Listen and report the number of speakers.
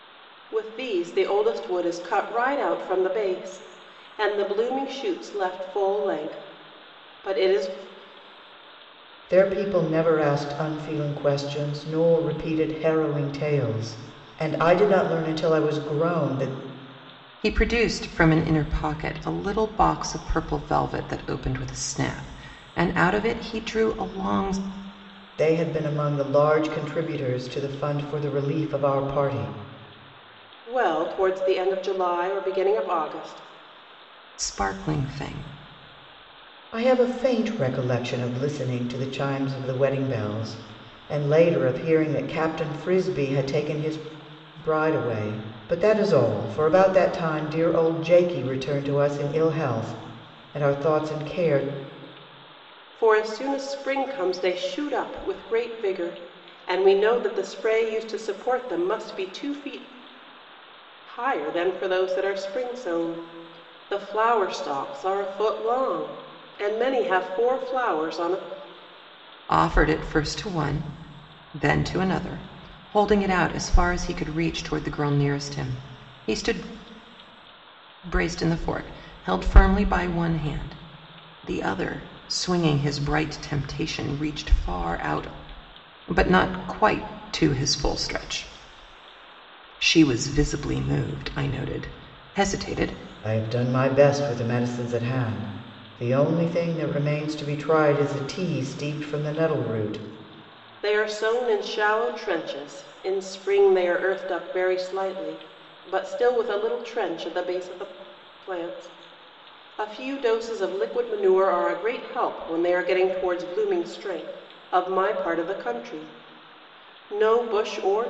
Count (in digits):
3